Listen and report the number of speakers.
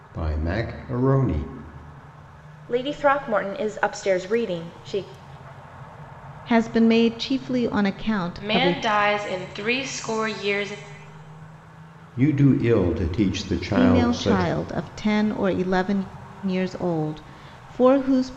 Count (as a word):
four